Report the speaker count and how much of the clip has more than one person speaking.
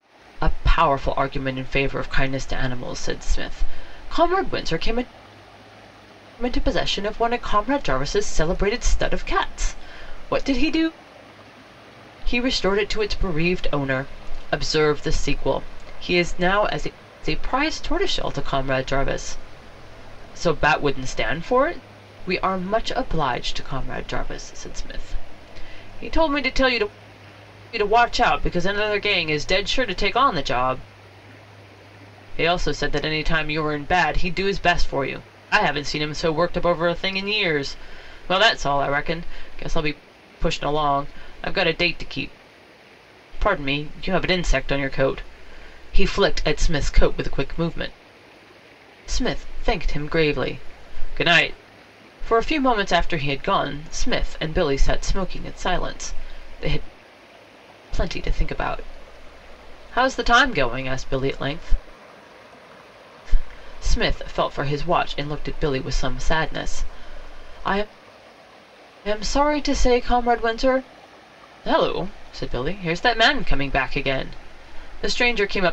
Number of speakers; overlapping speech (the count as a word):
one, no overlap